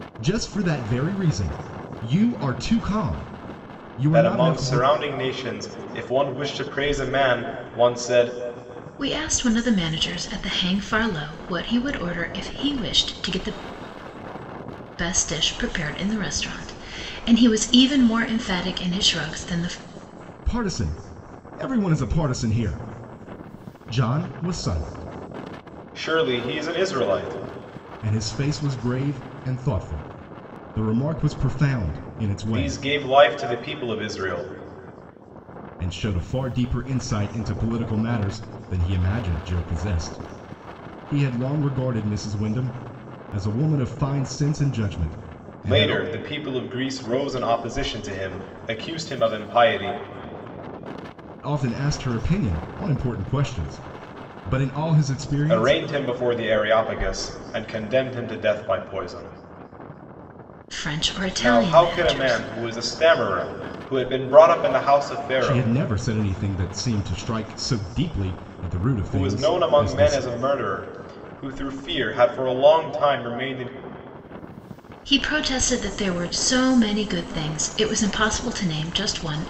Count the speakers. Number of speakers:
three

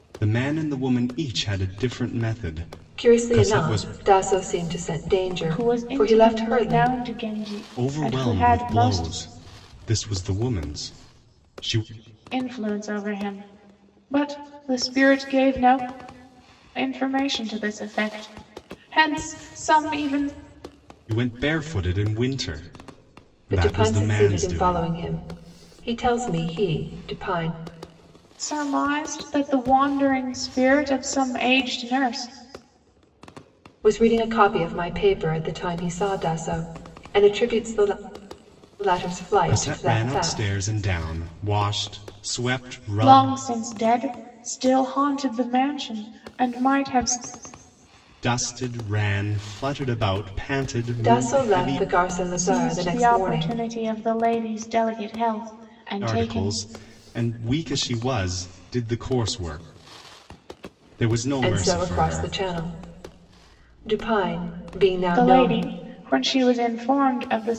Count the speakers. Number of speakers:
three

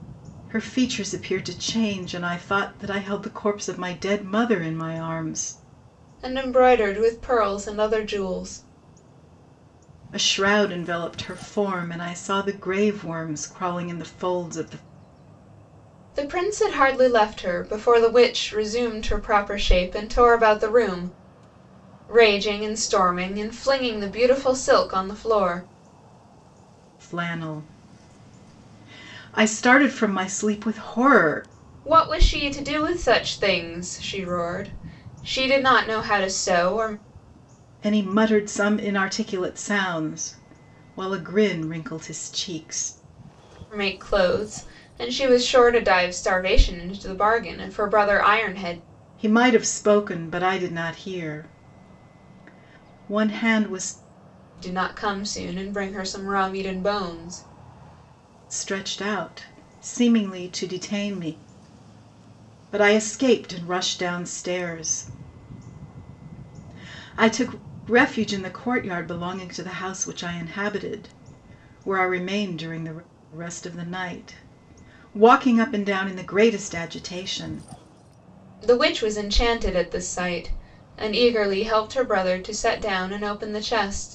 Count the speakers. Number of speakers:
two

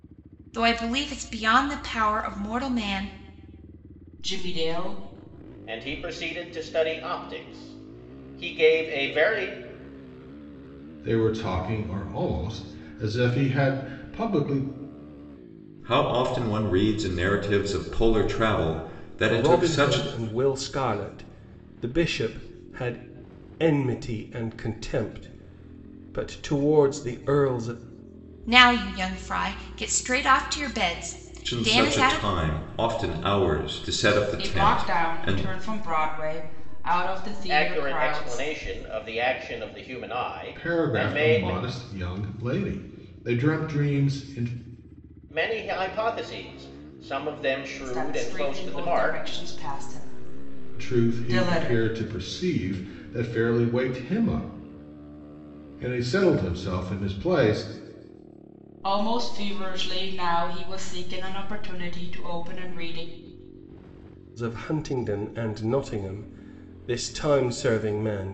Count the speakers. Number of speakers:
six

